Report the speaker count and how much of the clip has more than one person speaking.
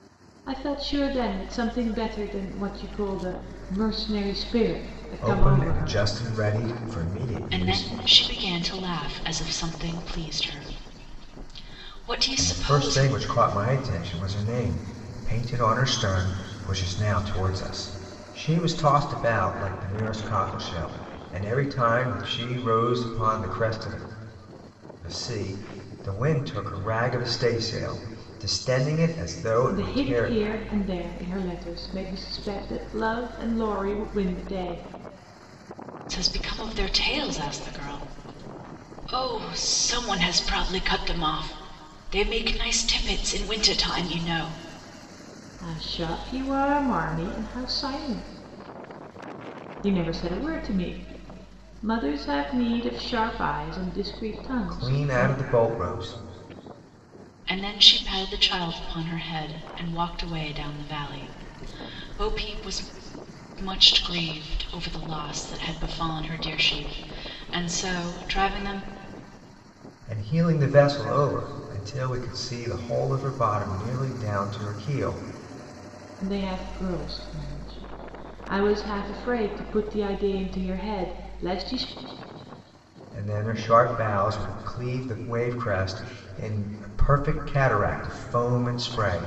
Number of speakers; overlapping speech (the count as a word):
three, about 4%